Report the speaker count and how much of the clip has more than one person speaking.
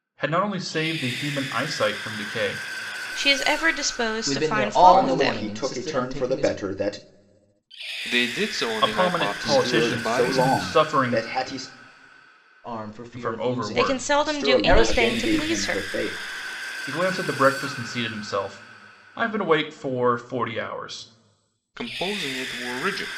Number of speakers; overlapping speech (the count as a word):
five, about 33%